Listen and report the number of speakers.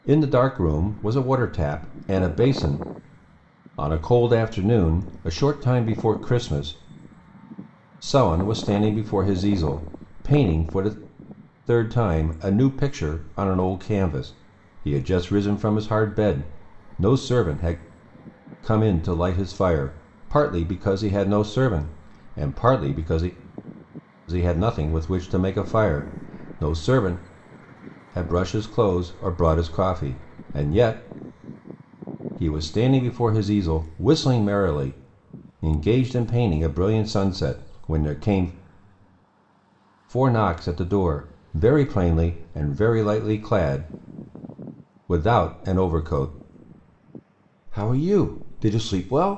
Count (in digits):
1